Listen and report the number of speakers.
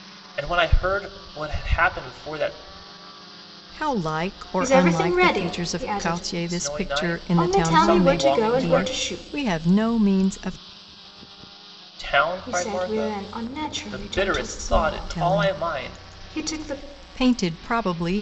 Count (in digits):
3